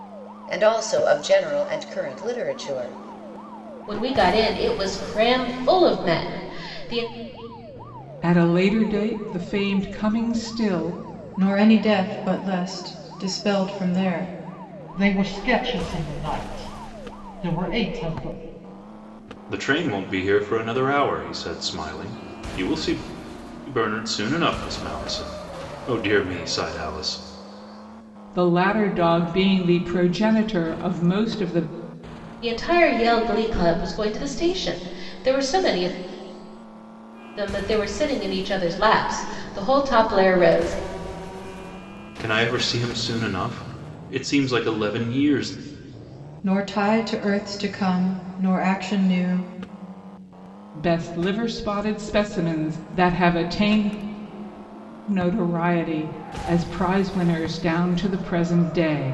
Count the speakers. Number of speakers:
6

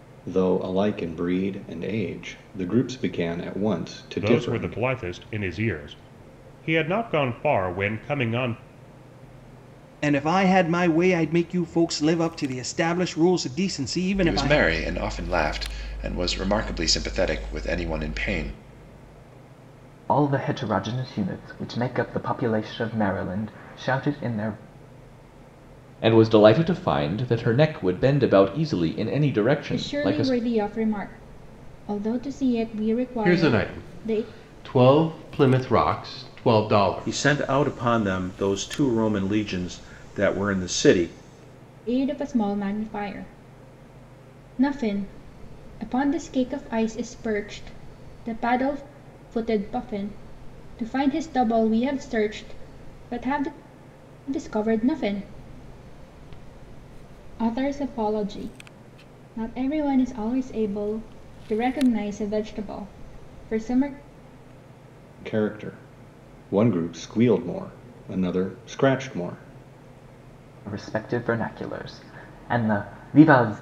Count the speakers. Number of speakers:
9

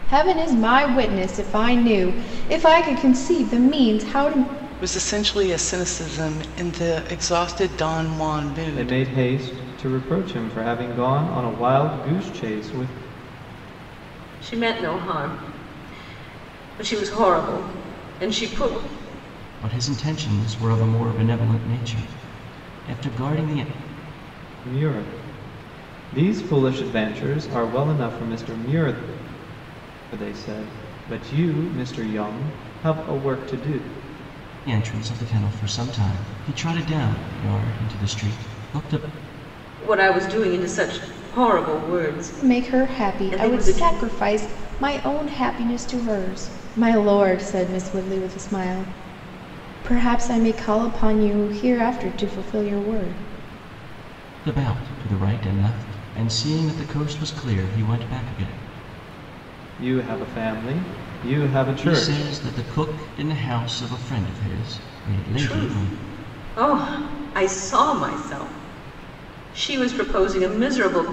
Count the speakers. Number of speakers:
5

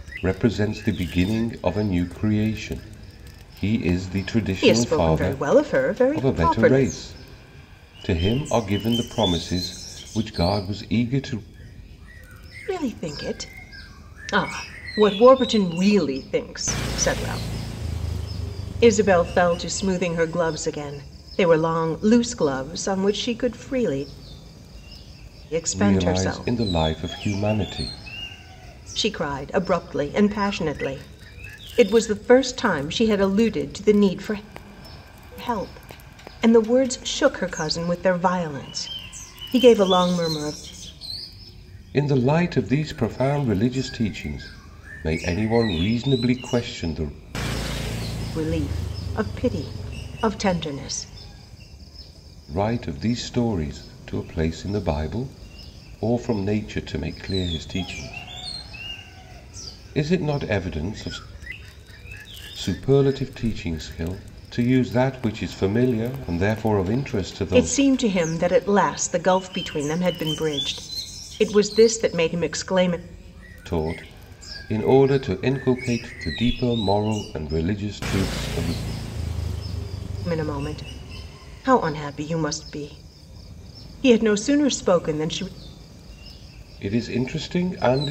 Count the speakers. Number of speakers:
2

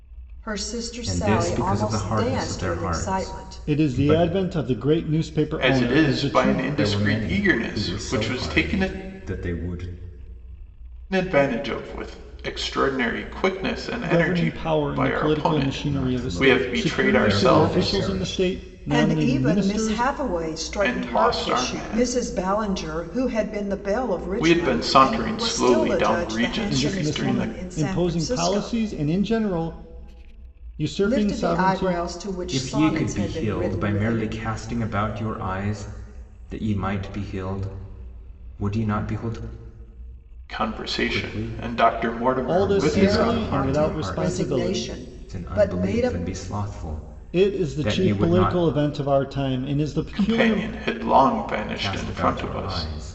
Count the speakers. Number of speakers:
4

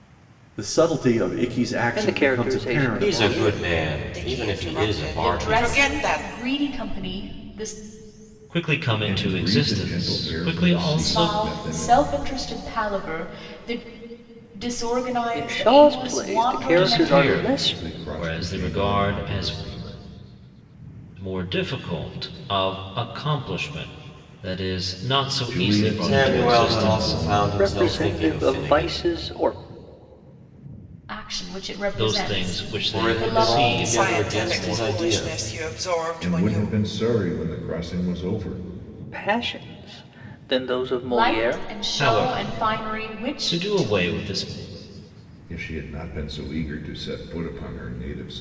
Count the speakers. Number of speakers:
7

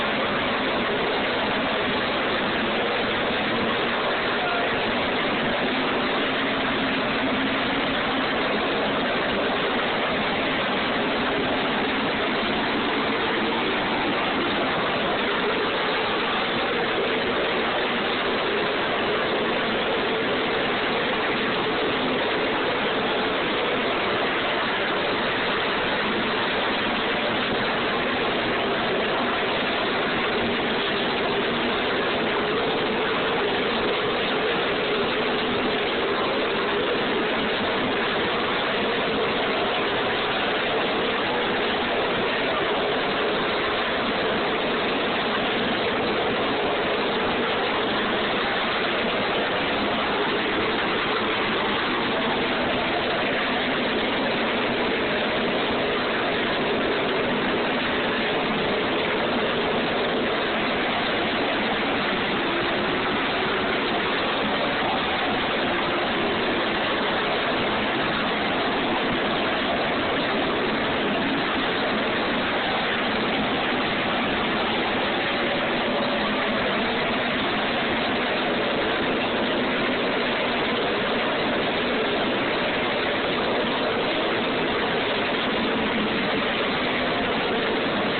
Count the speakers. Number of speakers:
0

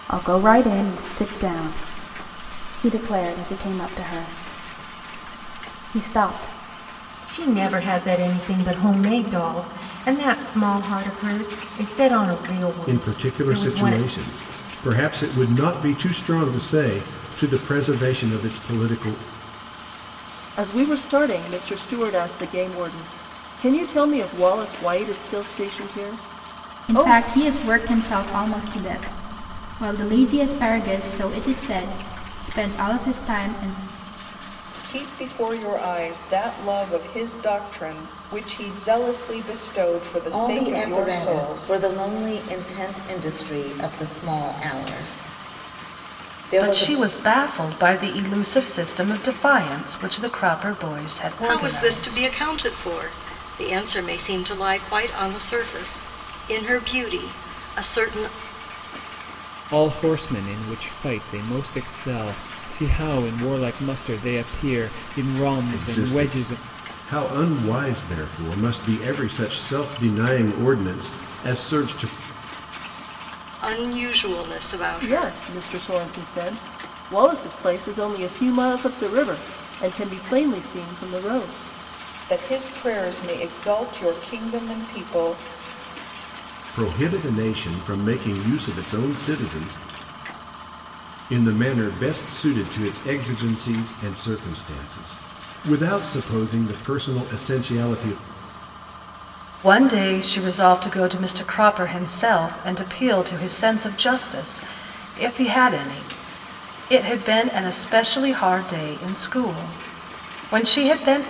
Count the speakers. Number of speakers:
10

